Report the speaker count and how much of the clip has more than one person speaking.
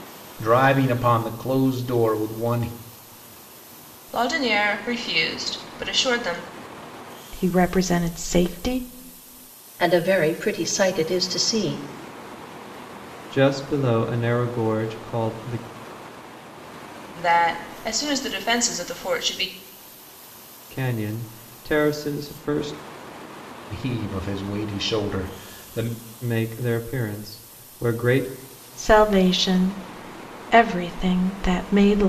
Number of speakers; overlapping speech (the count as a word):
five, no overlap